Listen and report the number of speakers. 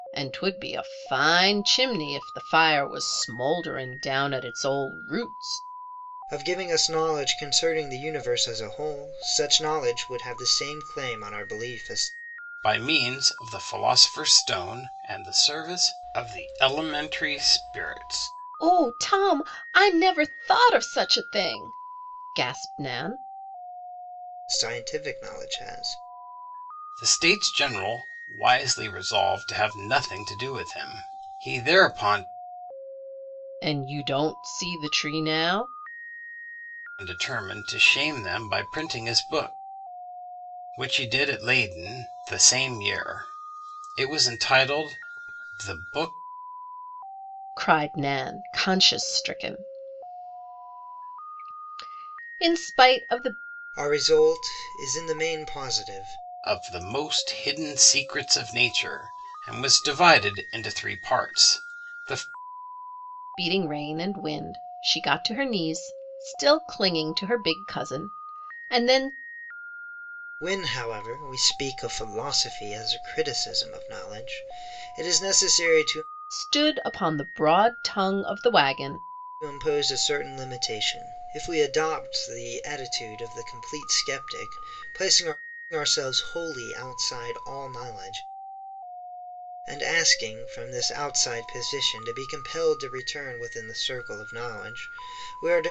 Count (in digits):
3